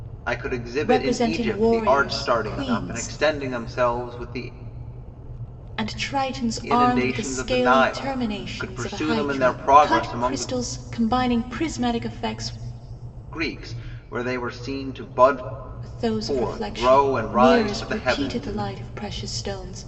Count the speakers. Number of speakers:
two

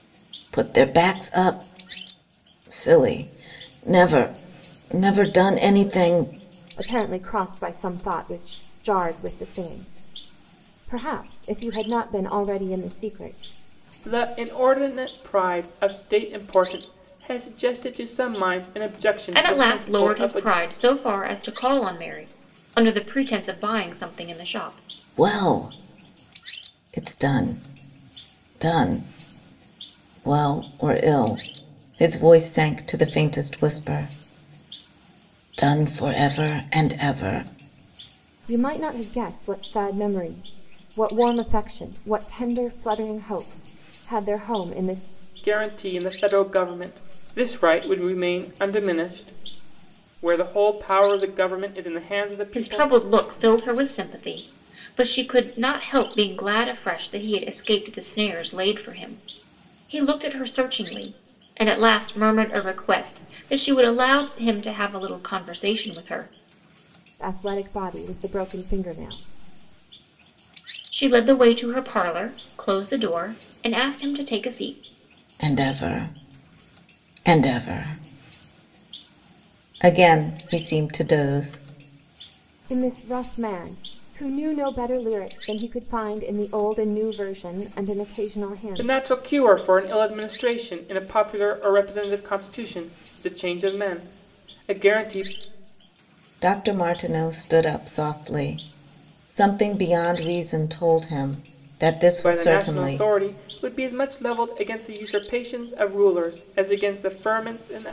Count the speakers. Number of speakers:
four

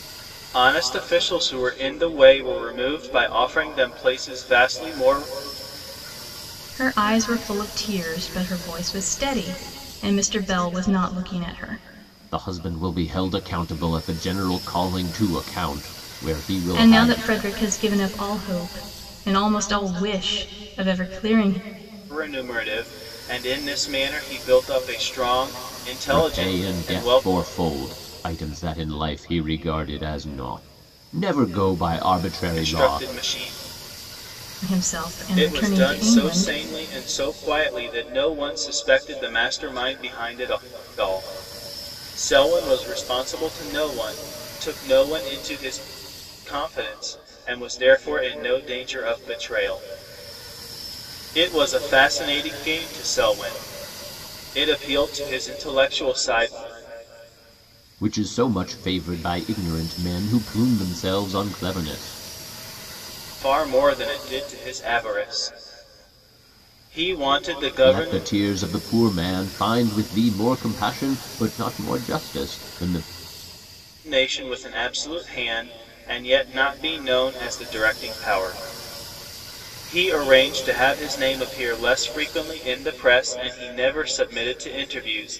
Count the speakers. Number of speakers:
three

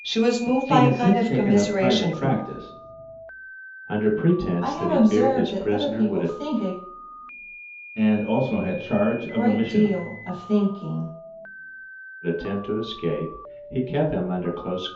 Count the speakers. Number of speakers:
four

